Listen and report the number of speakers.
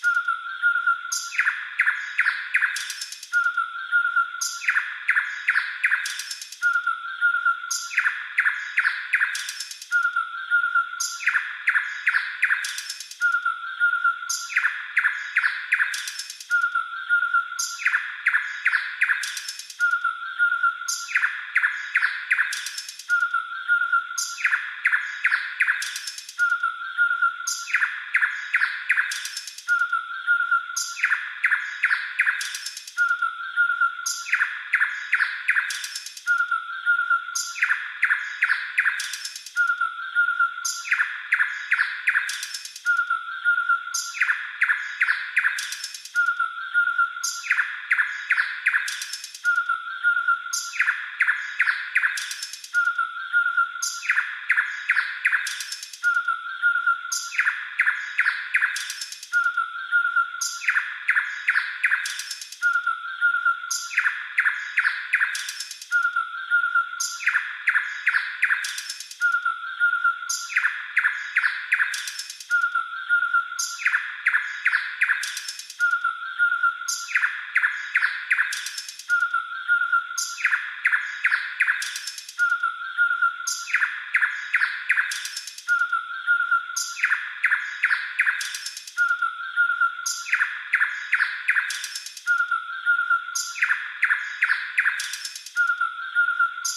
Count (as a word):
zero